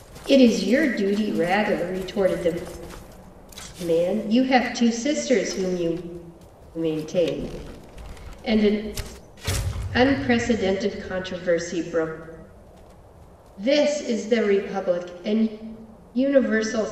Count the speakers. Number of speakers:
one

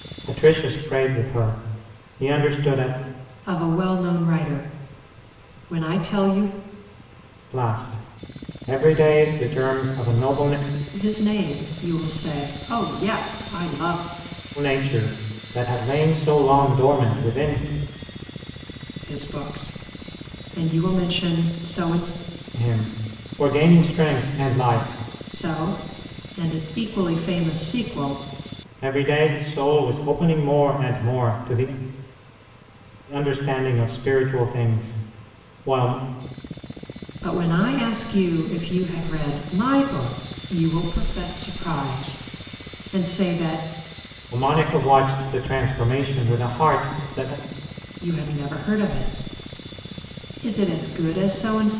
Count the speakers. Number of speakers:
two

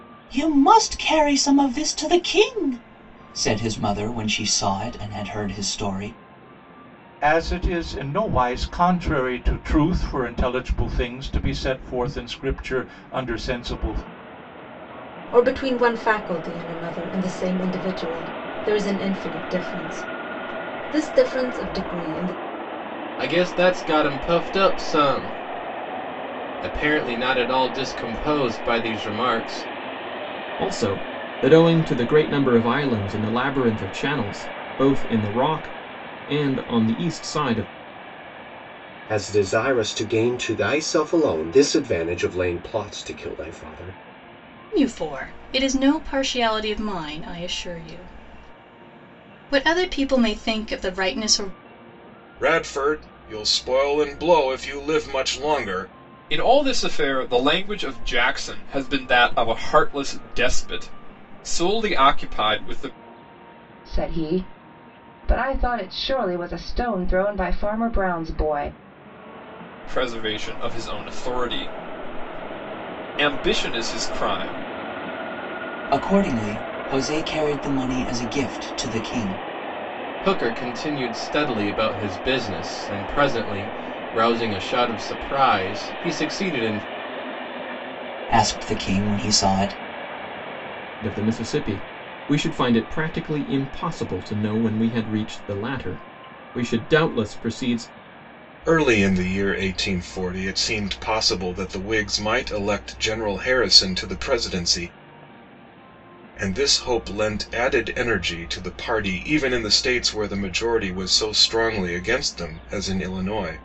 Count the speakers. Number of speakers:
ten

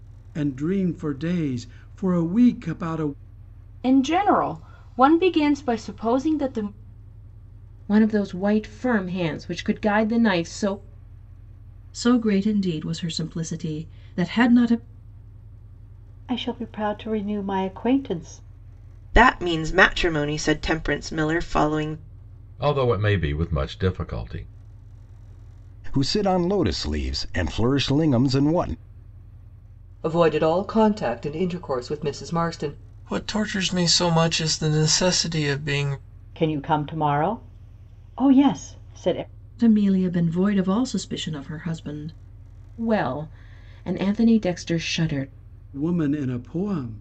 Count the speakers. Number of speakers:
ten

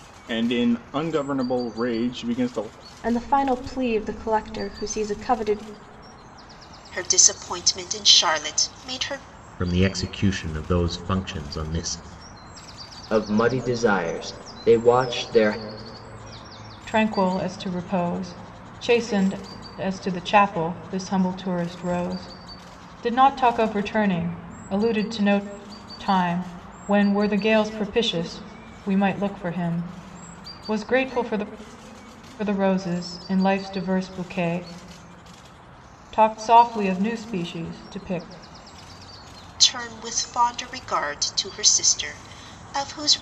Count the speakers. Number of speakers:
six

